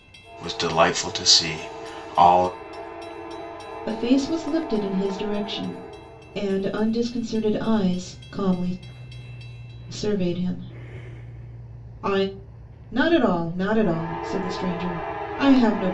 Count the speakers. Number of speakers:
2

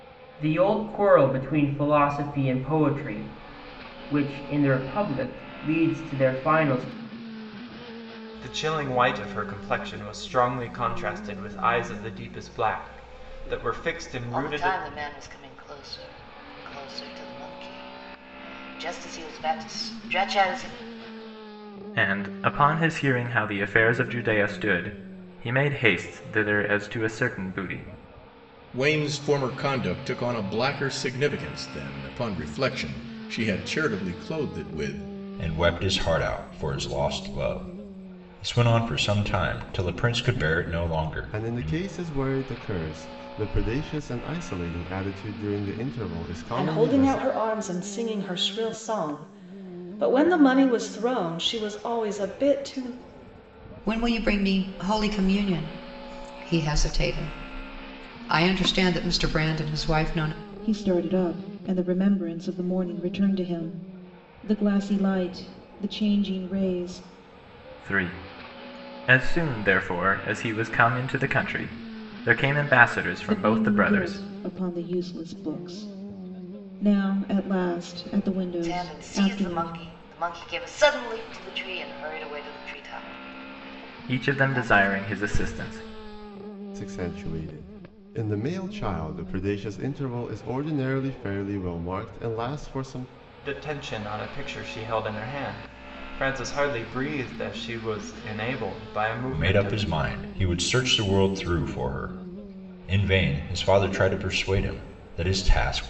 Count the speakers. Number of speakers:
10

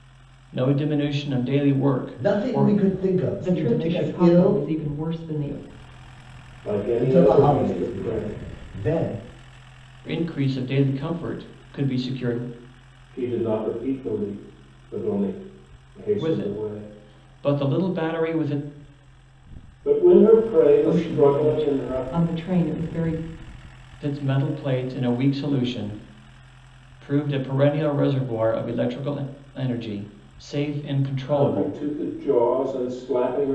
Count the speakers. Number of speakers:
4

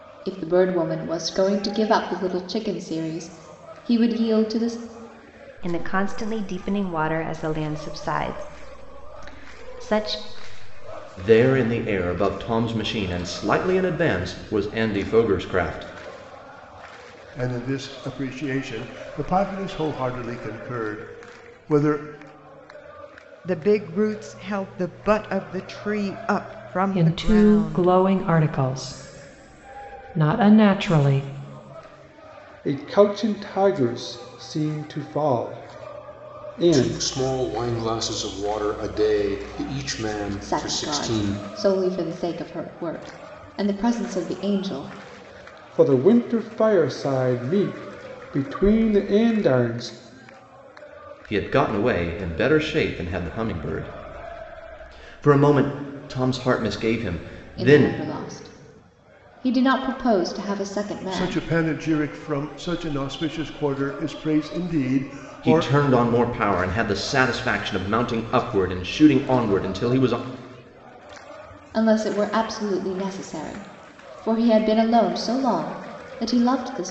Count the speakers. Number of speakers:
8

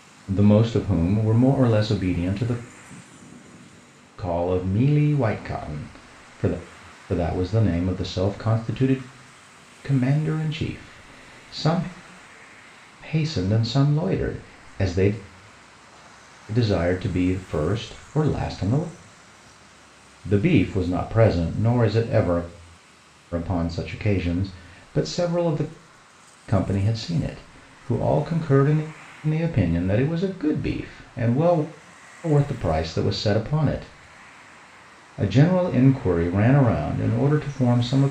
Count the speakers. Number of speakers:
1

